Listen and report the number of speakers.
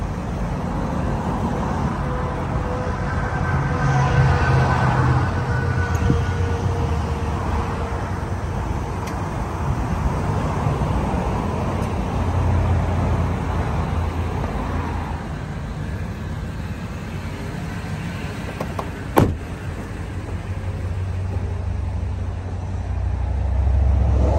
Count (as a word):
zero